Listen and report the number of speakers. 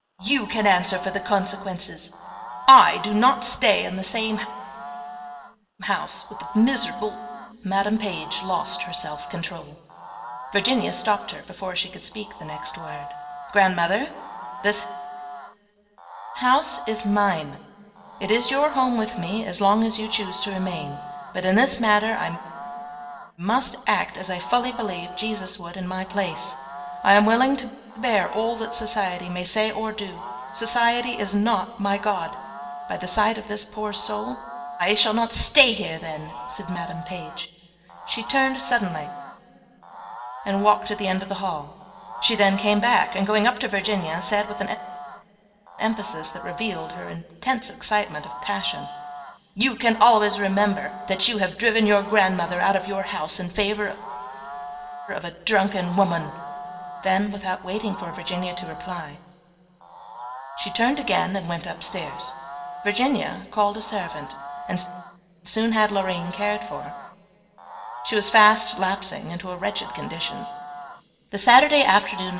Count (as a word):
one